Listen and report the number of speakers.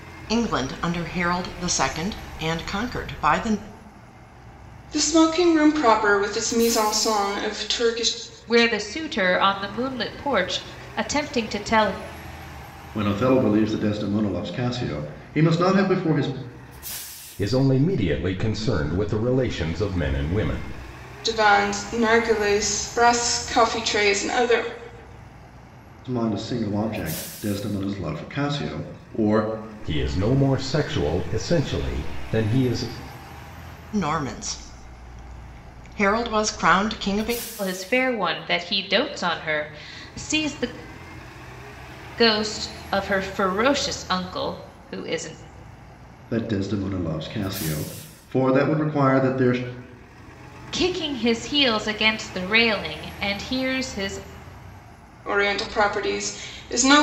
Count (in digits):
5